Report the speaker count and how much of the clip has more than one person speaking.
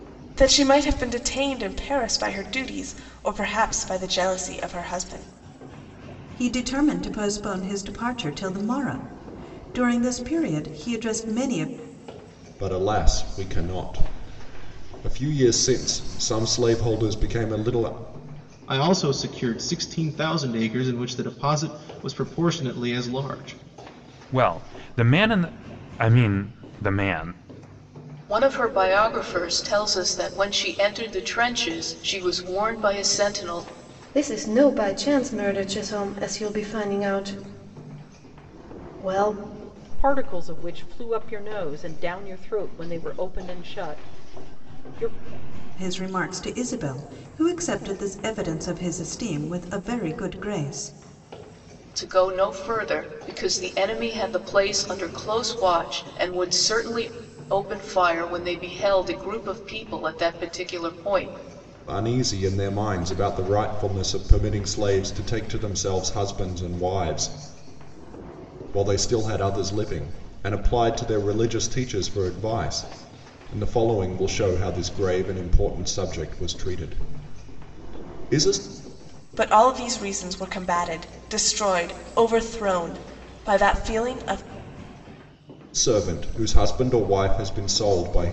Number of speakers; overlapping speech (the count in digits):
8, no overlap